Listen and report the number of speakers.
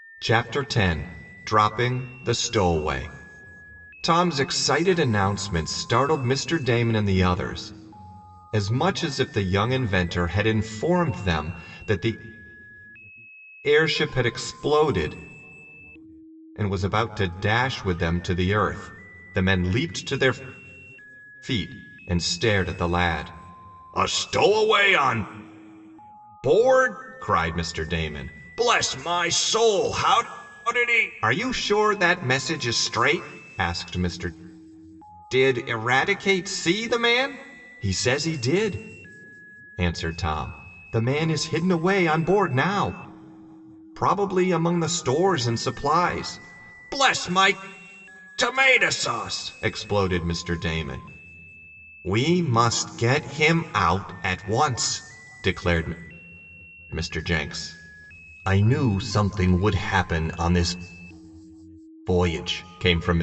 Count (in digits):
1